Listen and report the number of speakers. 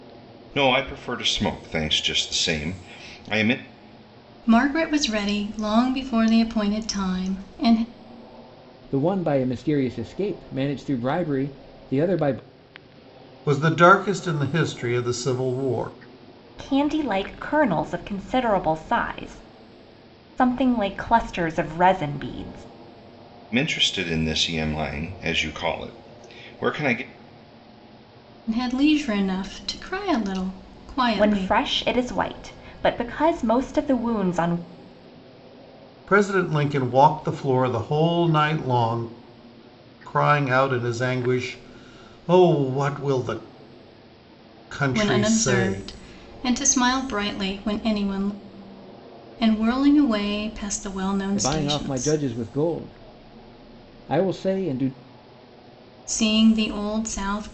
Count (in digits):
5